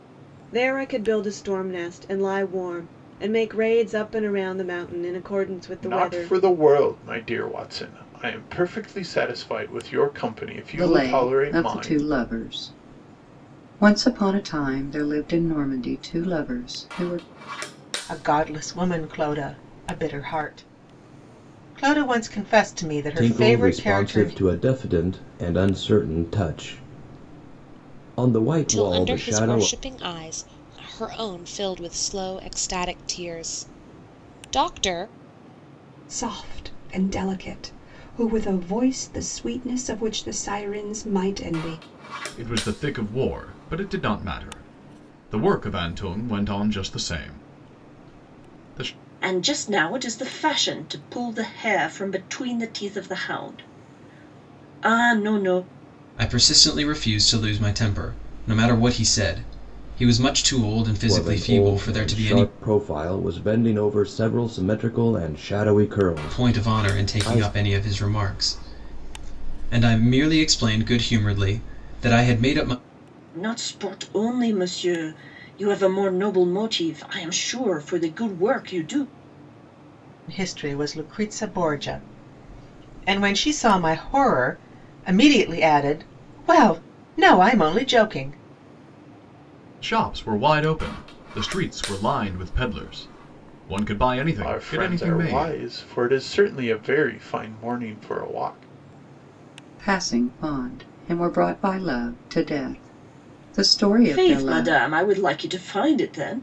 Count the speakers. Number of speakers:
ten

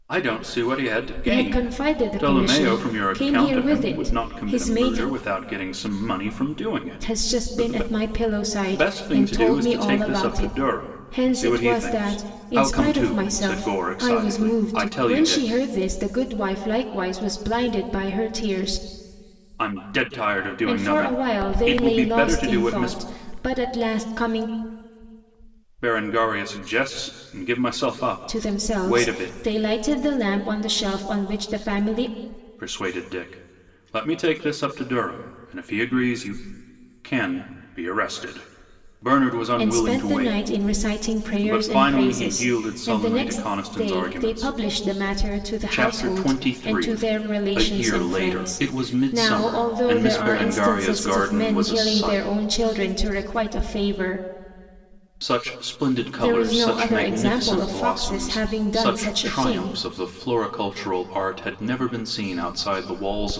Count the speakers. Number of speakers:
two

